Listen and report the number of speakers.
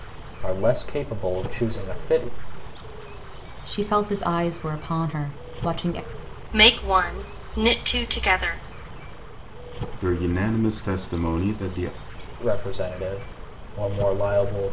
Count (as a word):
four